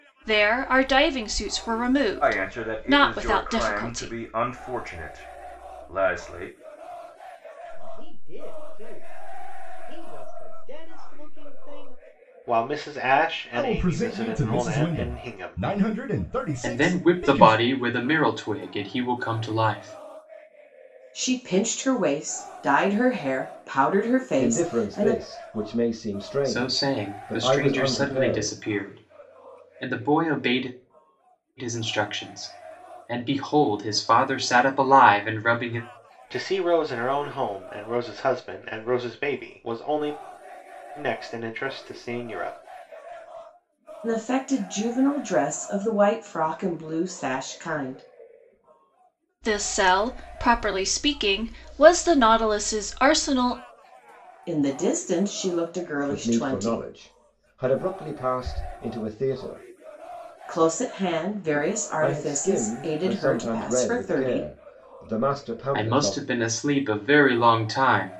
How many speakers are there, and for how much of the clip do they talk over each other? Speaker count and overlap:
eight, about 17%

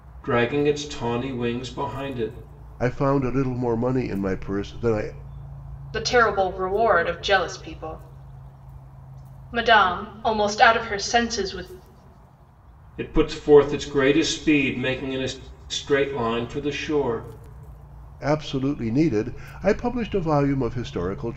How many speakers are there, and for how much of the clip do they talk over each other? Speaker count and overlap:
three, no overlap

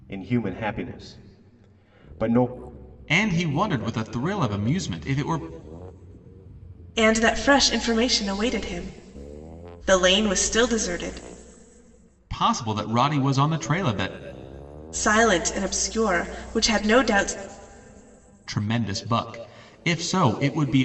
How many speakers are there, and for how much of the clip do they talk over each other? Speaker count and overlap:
three, no overlap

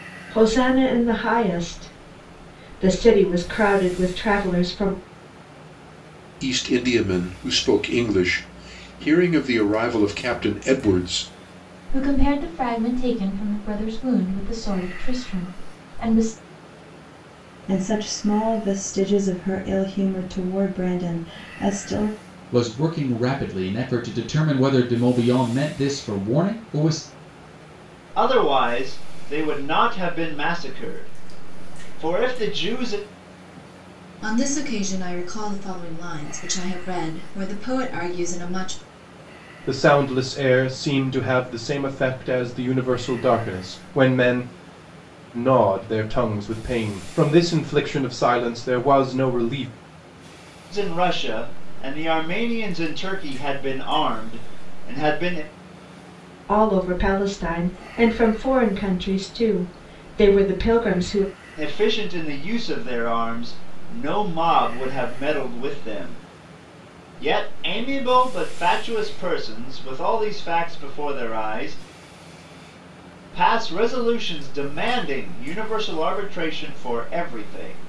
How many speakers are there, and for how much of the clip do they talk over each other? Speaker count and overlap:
eight, no overlap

